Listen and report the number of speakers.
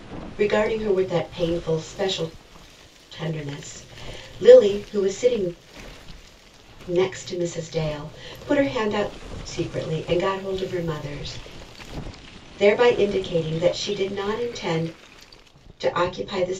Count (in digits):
1